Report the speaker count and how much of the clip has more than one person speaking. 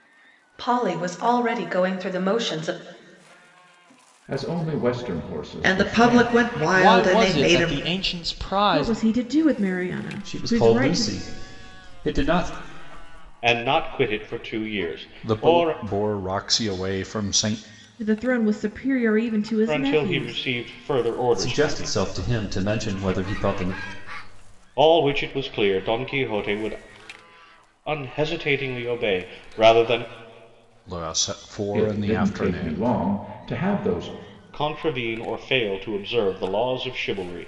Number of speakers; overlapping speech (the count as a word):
eight, about 17%